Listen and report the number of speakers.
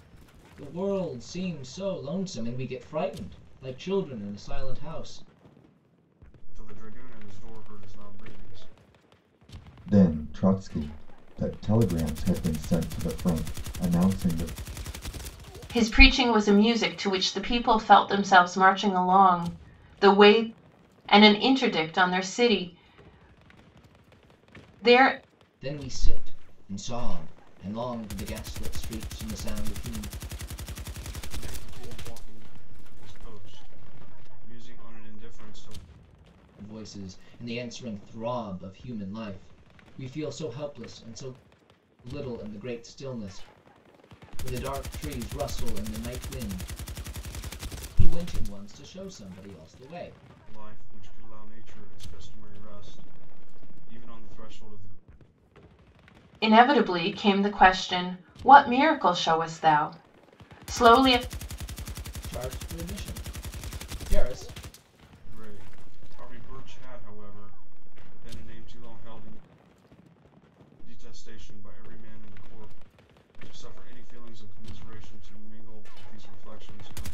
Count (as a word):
four